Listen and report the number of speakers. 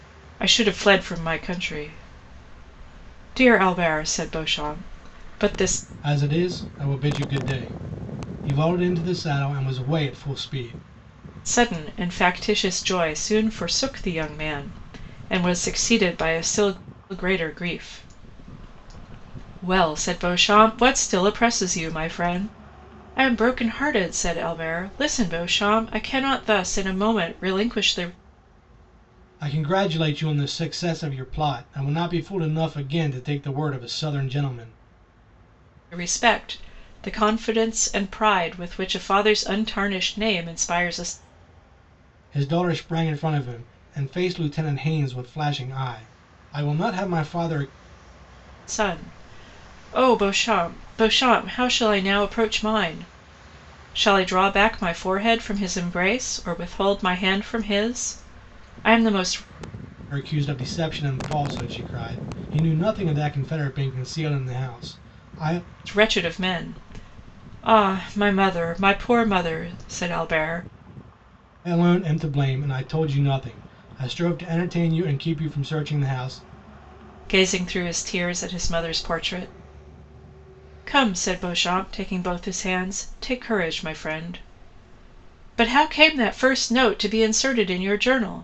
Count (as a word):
two